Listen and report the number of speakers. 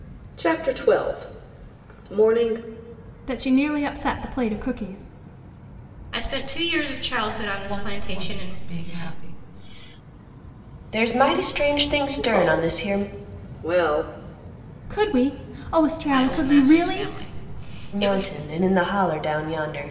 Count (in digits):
5